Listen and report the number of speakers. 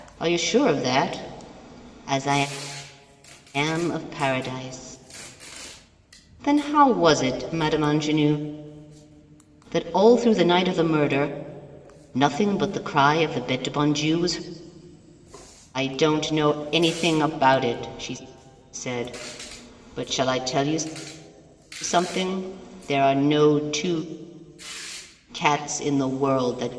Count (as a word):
one